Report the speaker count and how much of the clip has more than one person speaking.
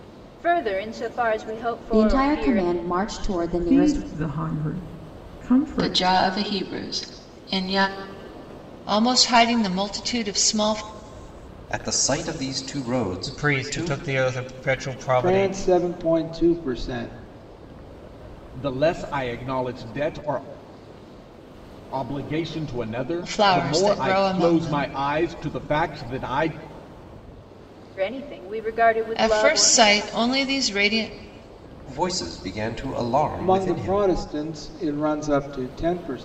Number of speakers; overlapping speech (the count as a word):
nine, about 17%